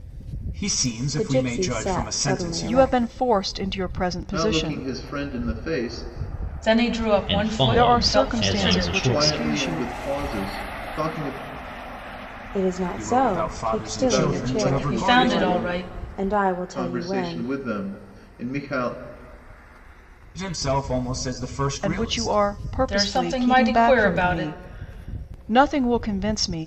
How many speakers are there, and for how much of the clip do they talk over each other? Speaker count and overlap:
six, about 44%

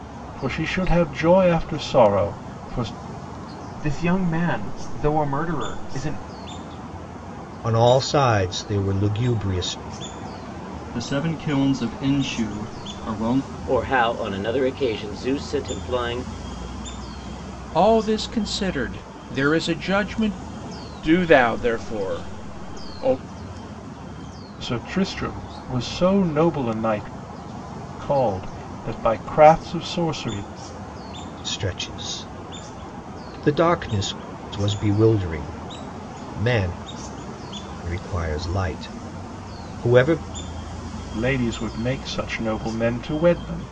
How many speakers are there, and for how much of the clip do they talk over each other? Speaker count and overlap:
seven, no overlap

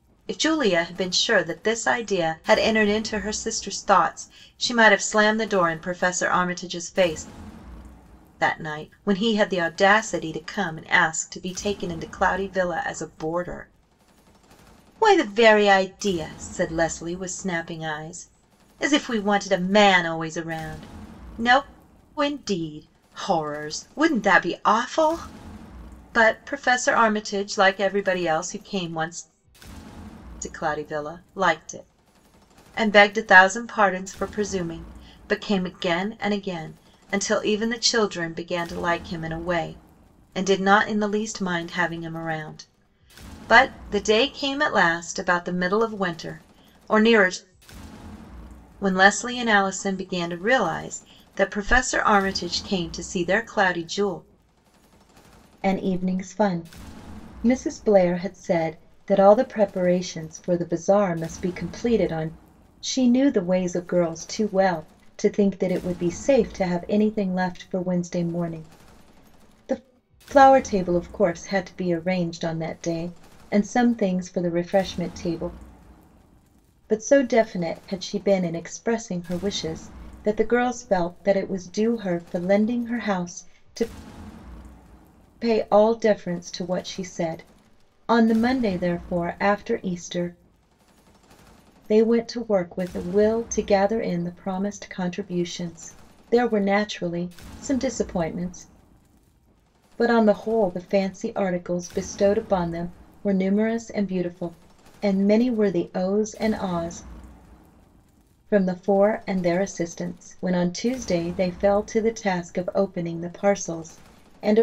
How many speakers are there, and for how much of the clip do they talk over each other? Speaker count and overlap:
one, no overlap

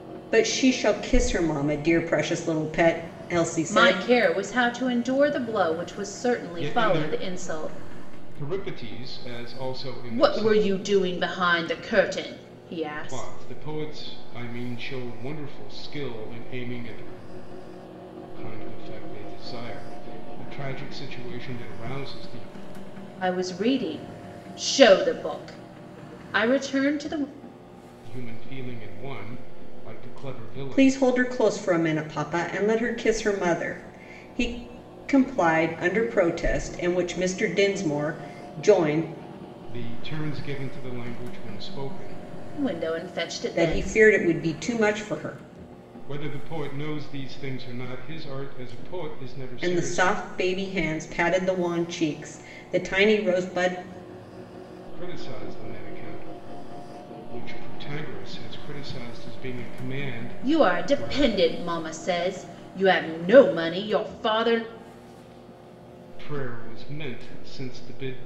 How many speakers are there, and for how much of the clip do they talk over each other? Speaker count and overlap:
three, about 8%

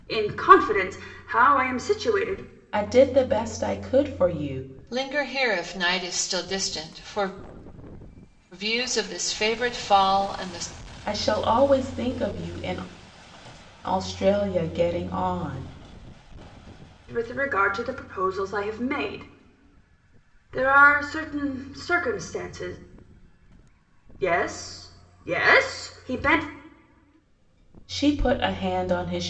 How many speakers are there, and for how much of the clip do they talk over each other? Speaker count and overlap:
three, no overlap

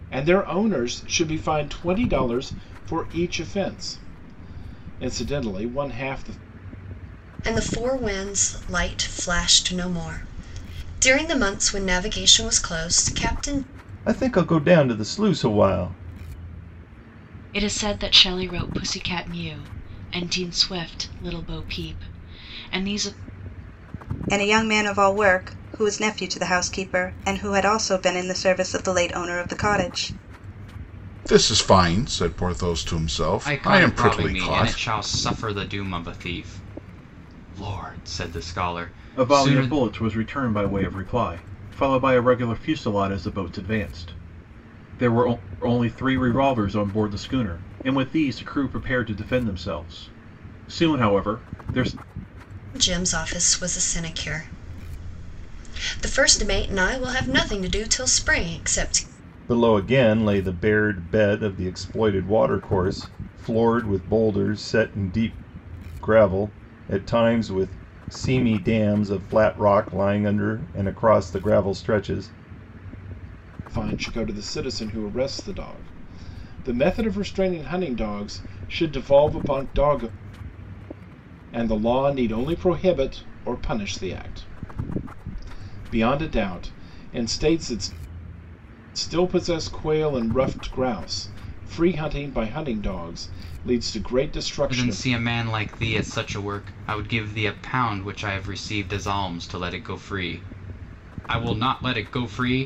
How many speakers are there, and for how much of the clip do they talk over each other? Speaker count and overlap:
eight, about 2%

